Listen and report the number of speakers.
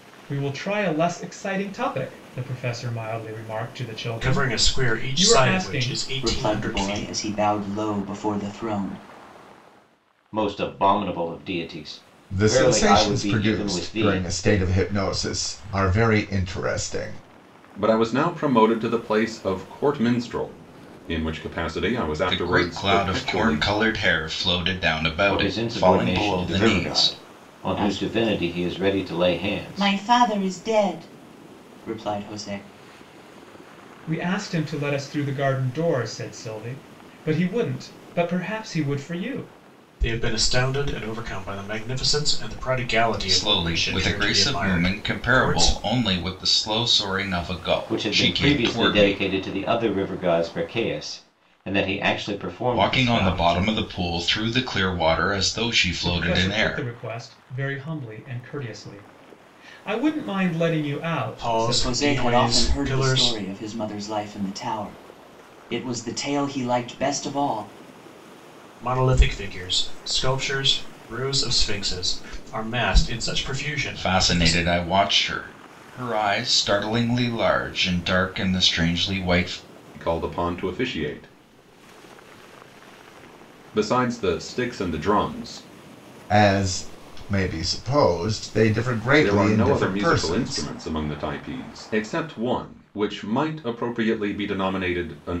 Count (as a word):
seven